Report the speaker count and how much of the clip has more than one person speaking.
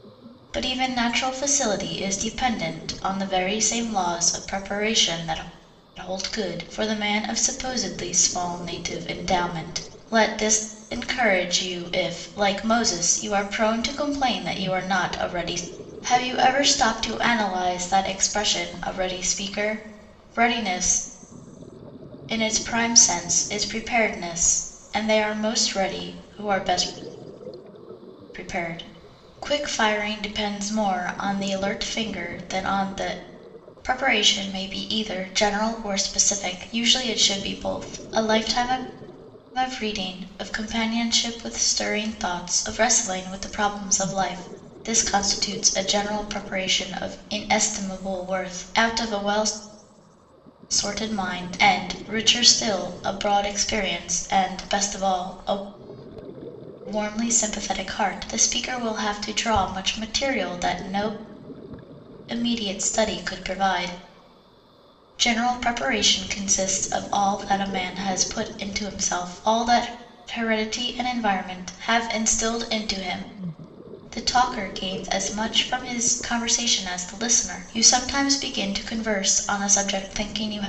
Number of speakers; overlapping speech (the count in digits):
1, no overlap